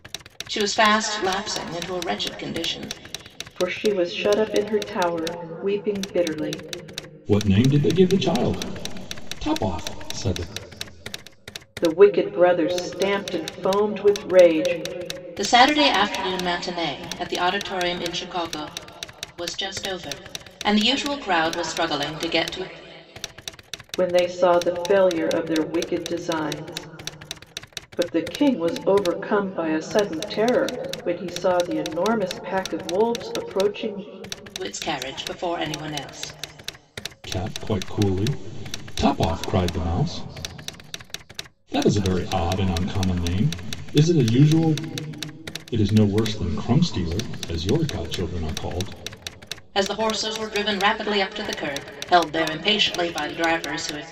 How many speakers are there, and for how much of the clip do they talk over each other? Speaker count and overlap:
three, no overlap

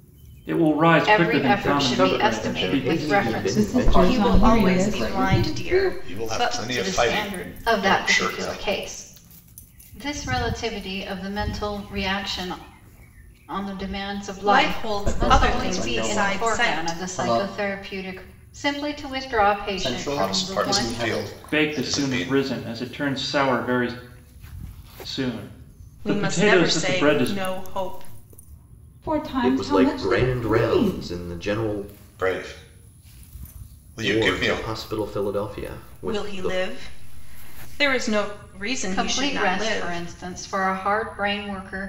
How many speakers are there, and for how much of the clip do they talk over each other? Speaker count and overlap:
seven, about 44%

